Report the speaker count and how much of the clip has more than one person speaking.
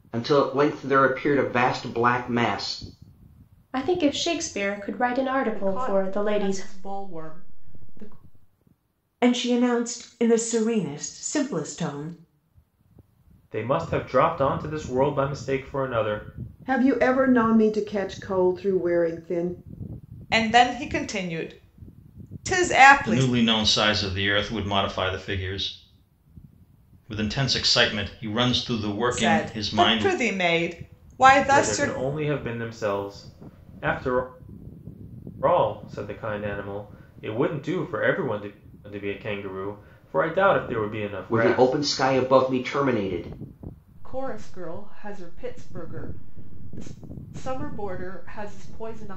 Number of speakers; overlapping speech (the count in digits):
8, about 7%